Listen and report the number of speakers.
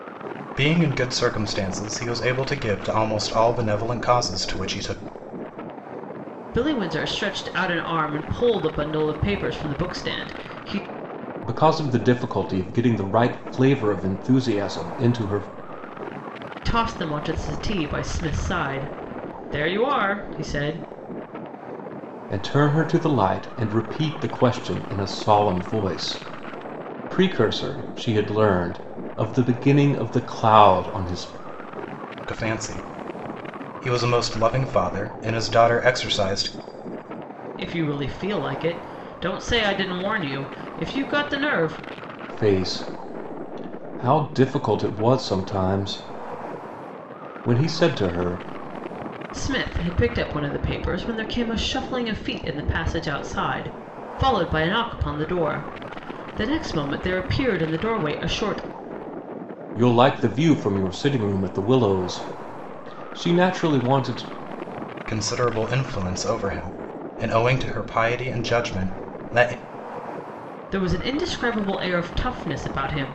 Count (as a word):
three